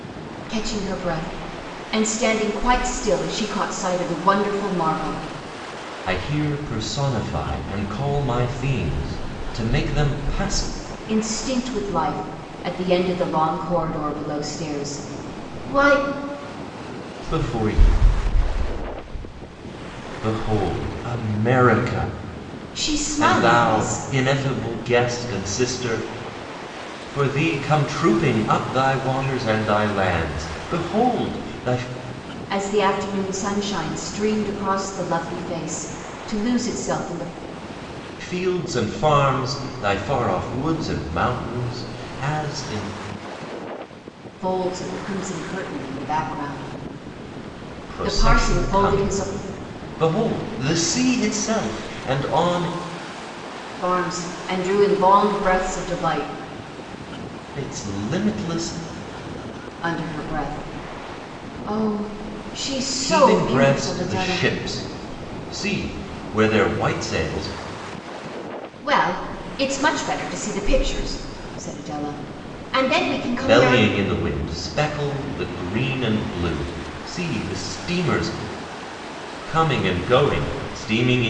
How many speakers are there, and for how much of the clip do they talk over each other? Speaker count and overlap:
two, about 5%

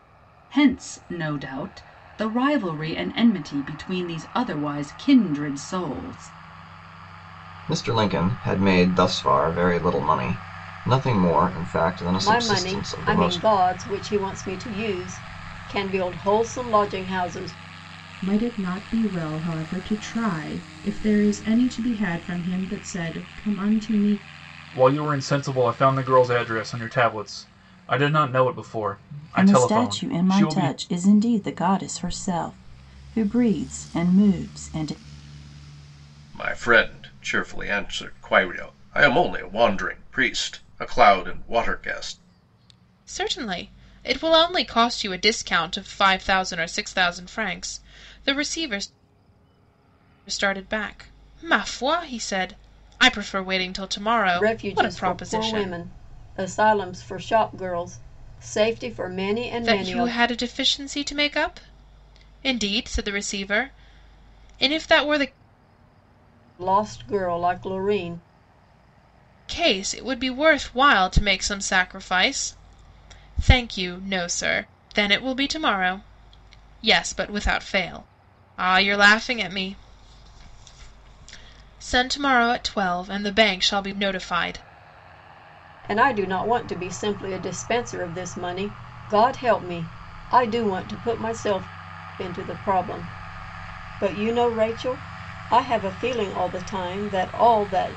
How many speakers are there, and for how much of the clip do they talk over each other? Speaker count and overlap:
eight, about 5%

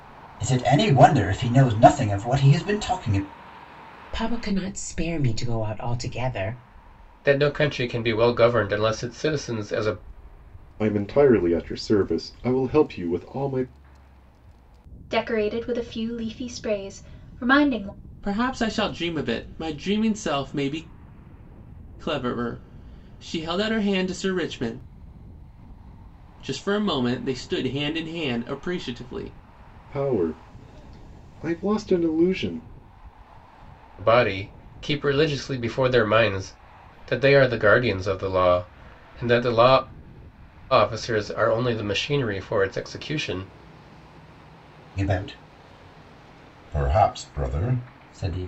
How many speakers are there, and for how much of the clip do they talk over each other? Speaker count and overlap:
six, no overlap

